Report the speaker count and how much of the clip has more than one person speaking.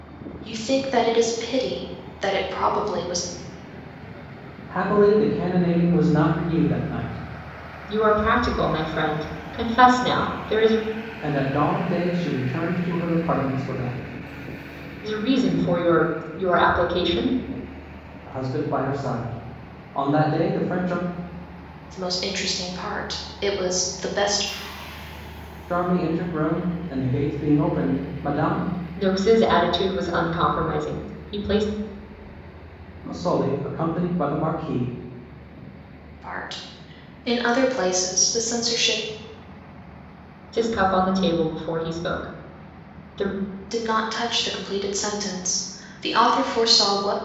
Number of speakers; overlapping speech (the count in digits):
3, no overlap